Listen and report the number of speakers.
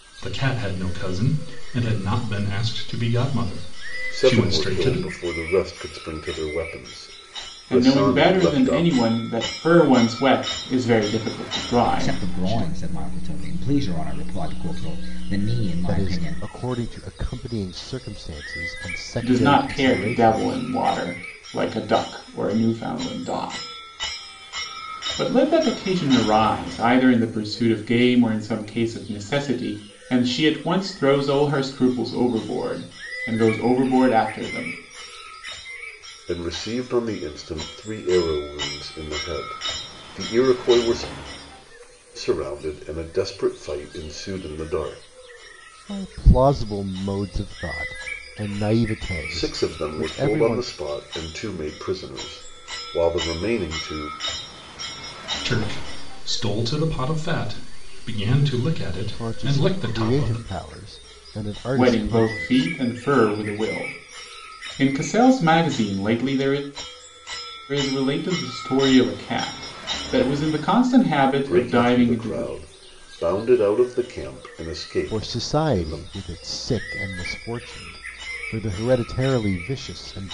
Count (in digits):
5